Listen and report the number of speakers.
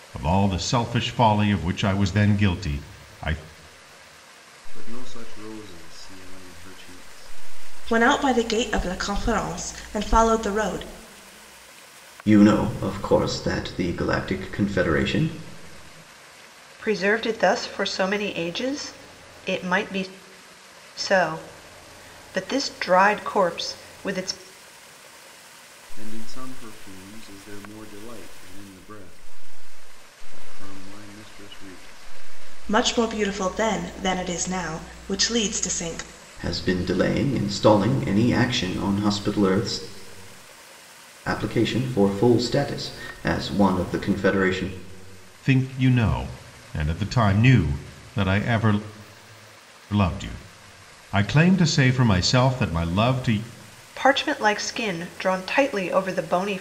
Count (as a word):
five